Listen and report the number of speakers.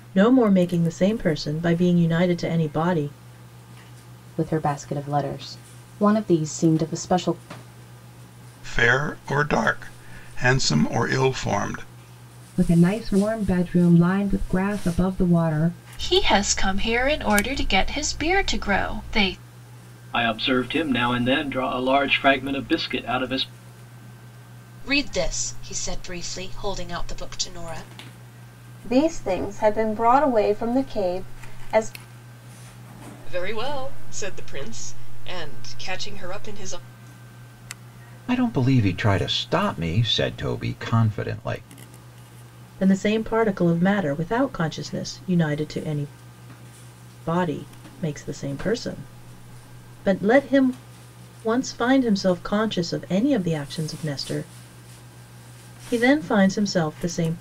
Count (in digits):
10